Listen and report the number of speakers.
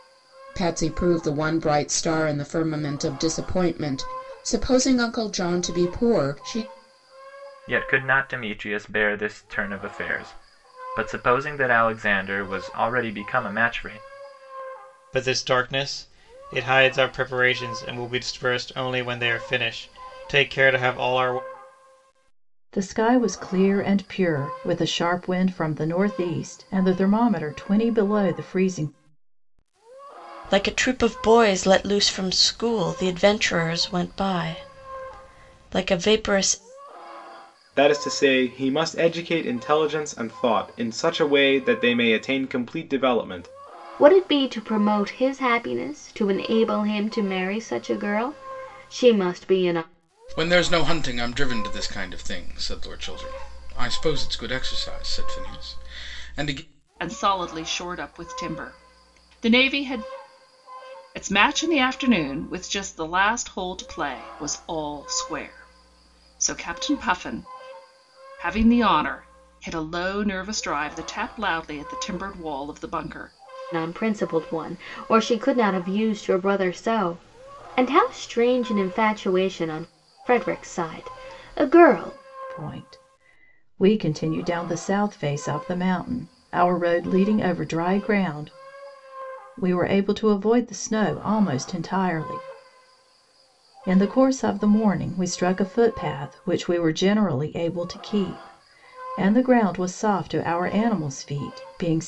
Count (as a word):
nine